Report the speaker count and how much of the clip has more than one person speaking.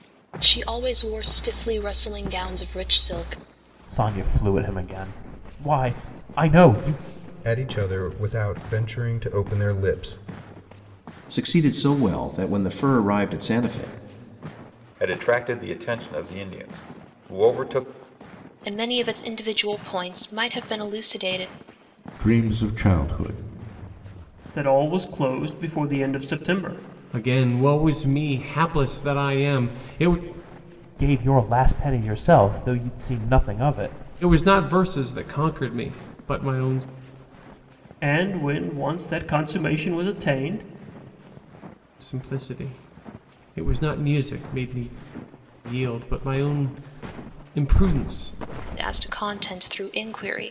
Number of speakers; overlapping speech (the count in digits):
9, no overlap